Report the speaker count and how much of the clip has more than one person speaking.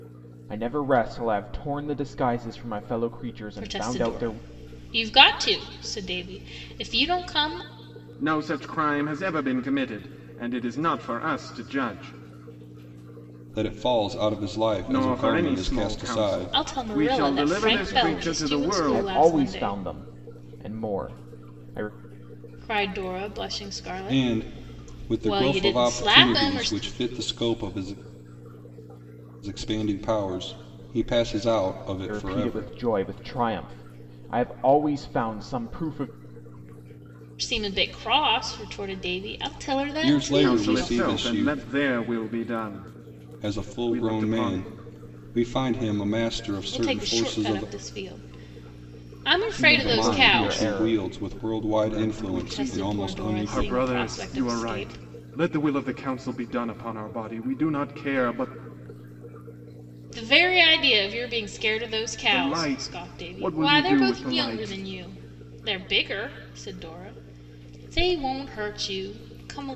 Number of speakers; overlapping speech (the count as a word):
four, about 29%